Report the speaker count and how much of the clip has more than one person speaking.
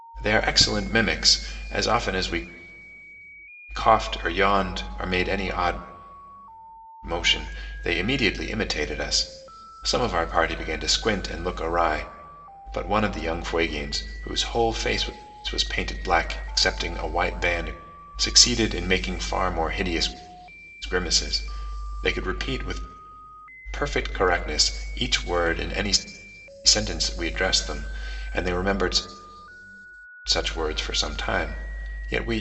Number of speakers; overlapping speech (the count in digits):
1, no overlap